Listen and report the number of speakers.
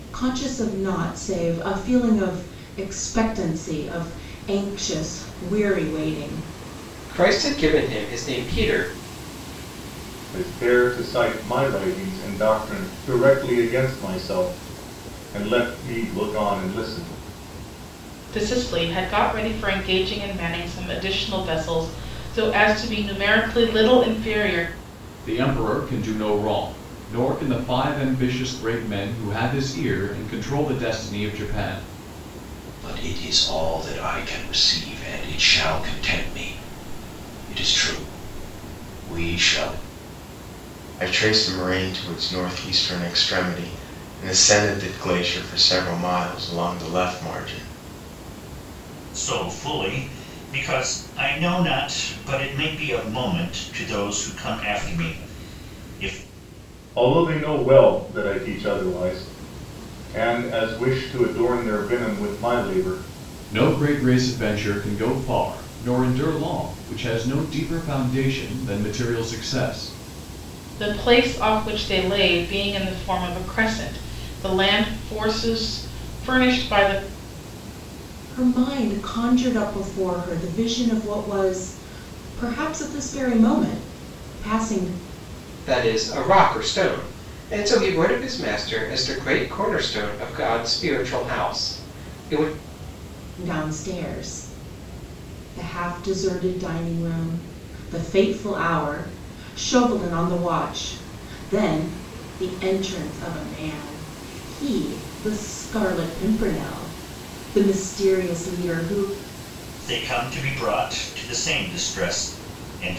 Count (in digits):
8